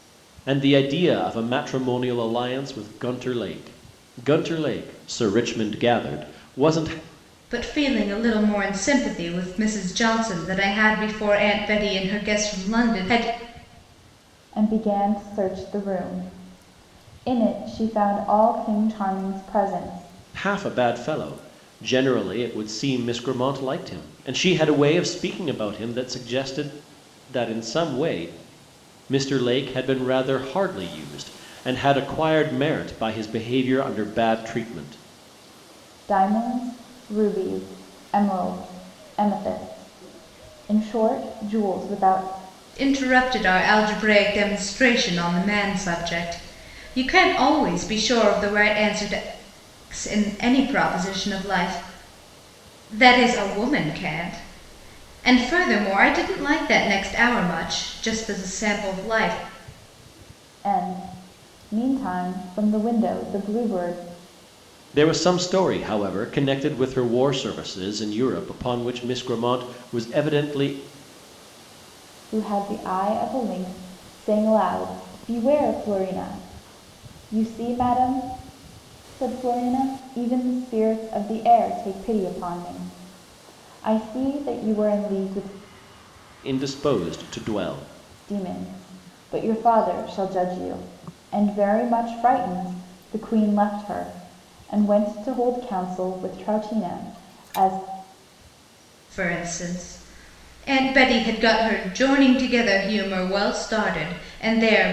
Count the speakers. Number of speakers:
three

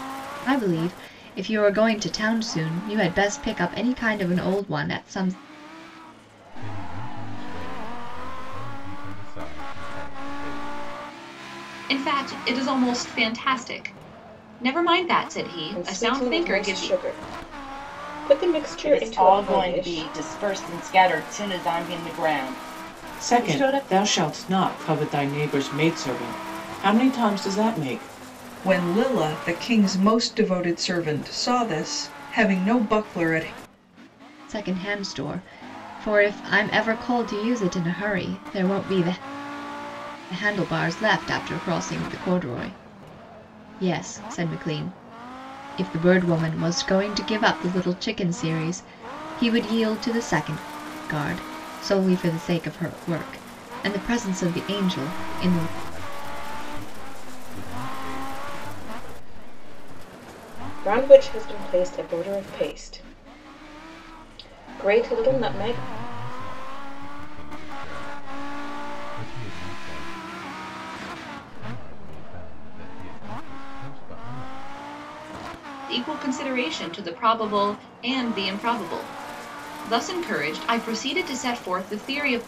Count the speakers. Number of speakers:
seven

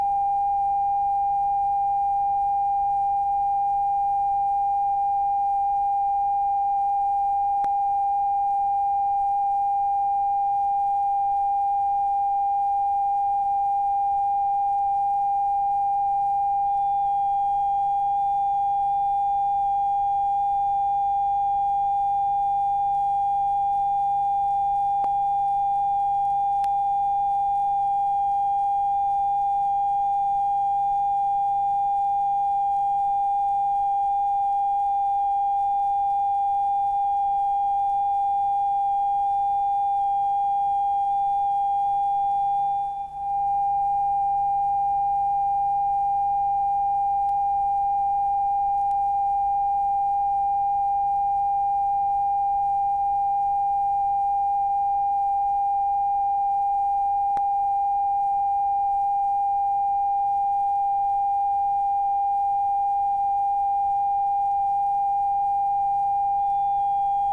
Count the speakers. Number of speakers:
zero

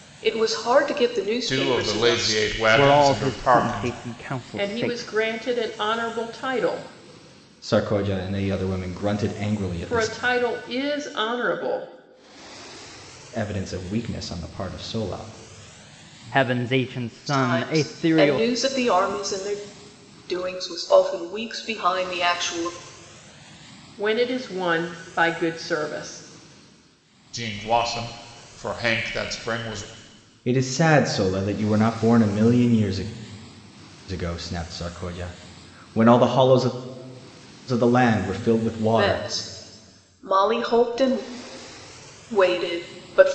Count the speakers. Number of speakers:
five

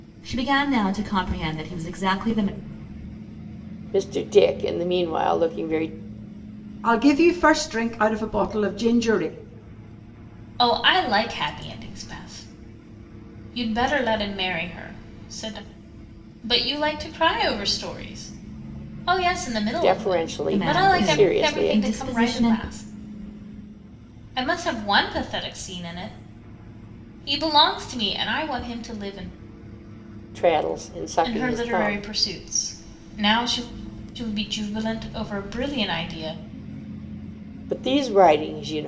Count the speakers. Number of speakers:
four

